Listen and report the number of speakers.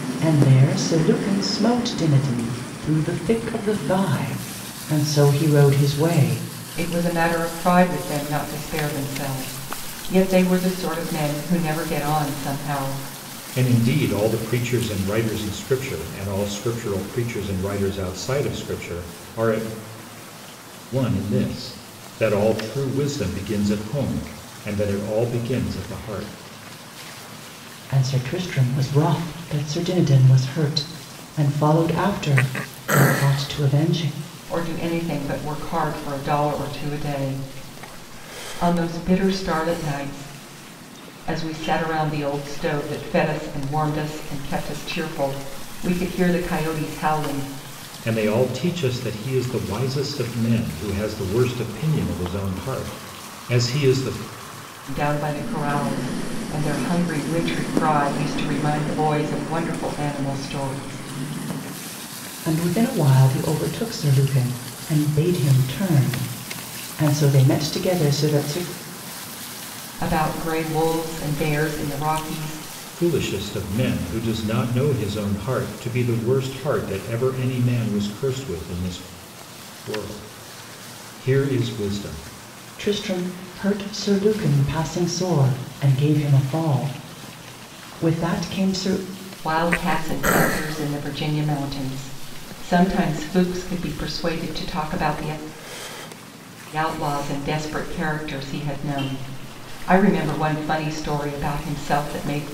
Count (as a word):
three